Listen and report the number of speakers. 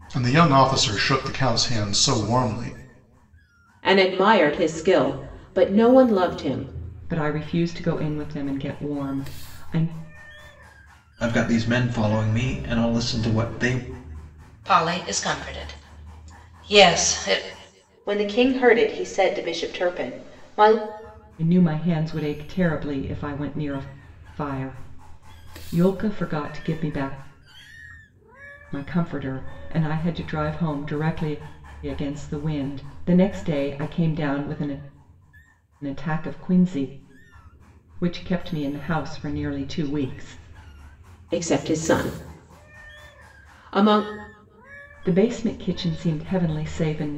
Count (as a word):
six